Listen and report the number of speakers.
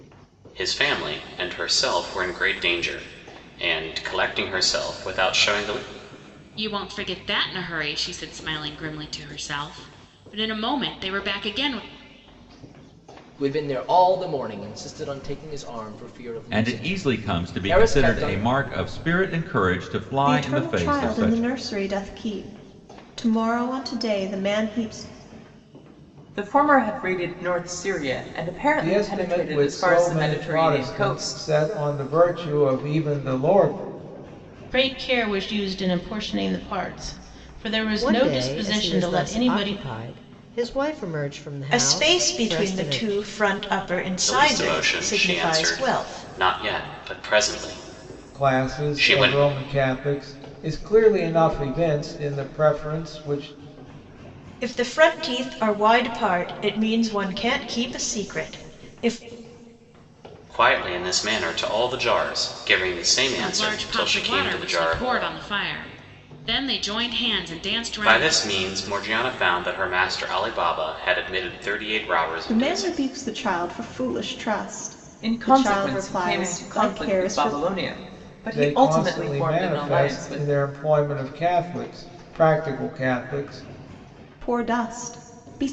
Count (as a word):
ten